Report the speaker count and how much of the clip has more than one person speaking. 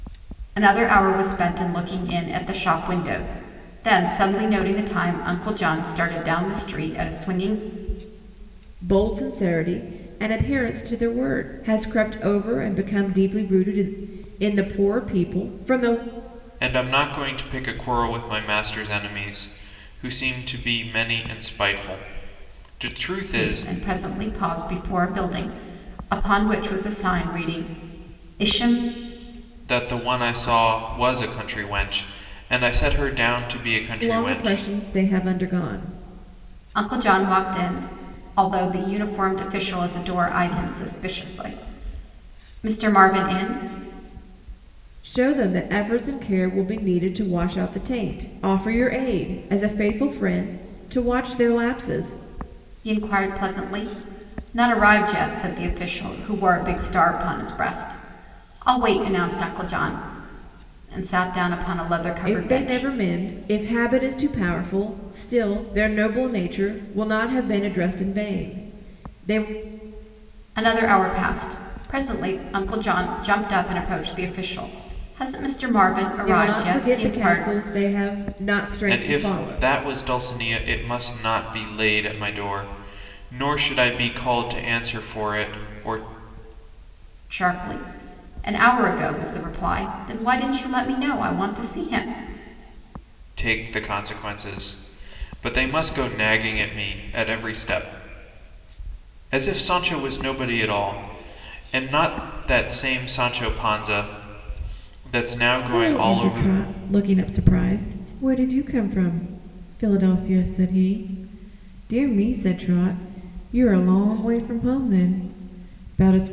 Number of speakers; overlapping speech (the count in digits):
3, about 4%